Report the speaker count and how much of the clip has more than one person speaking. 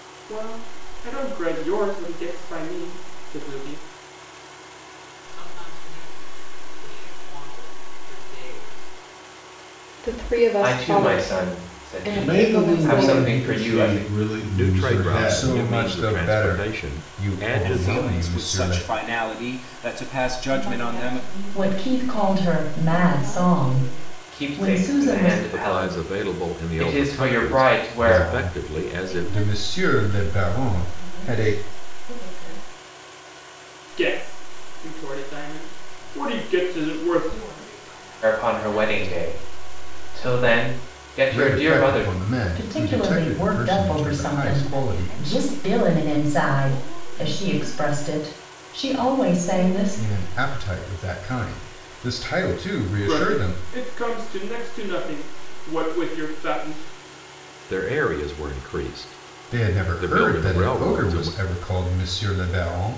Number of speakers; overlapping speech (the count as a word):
ten, about 54%